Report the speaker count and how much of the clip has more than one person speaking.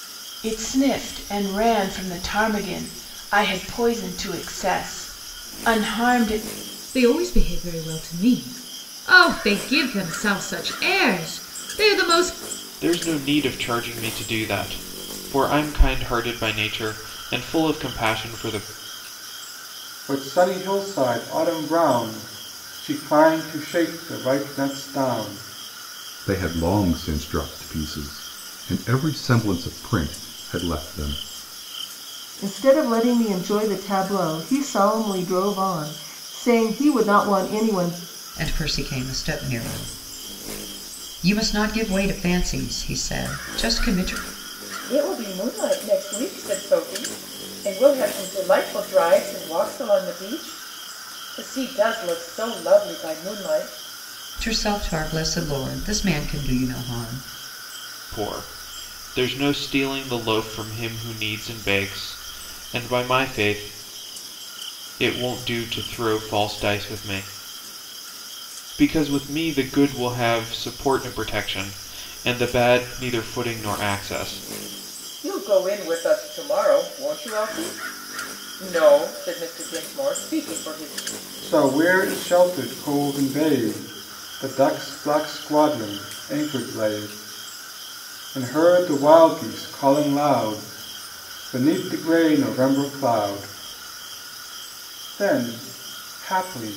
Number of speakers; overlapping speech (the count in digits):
8, no overlap